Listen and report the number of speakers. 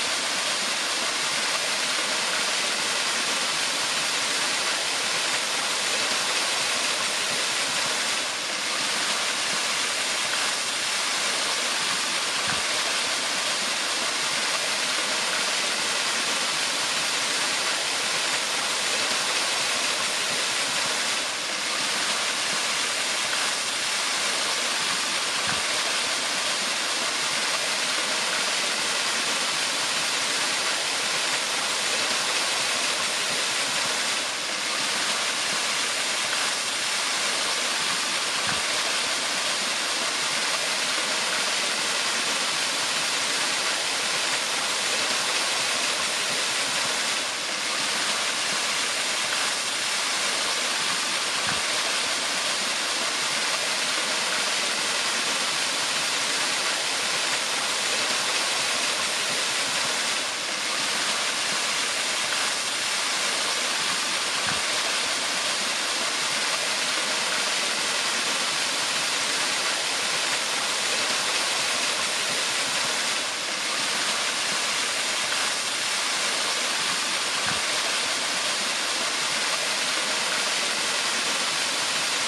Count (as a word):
zero